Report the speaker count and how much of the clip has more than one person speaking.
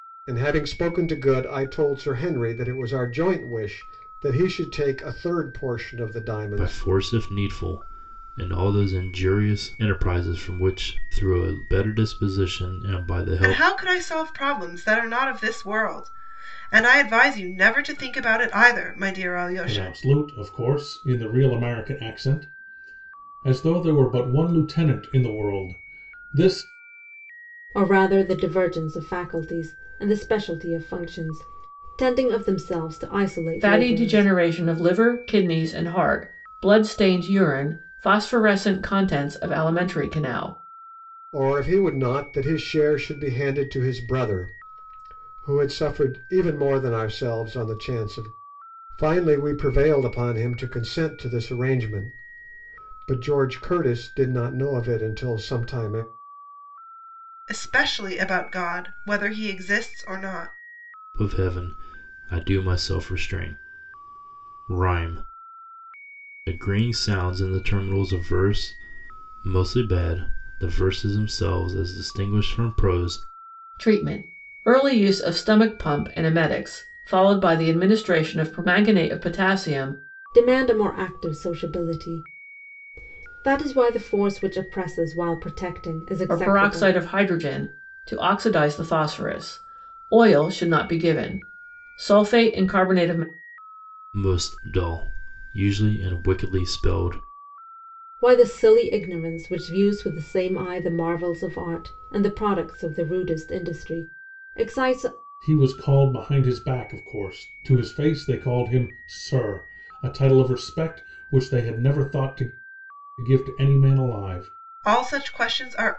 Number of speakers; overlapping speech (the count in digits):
6, about 2%